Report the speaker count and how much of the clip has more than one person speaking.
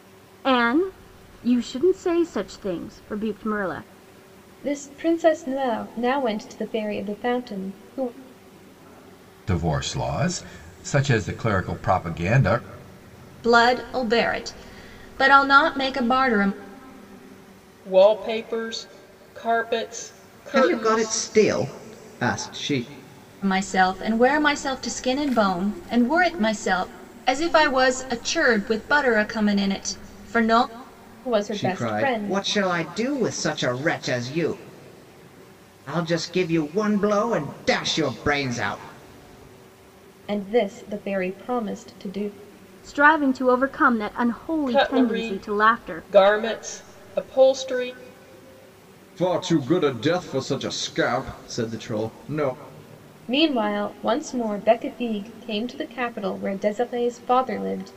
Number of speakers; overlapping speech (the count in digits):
6, about 5%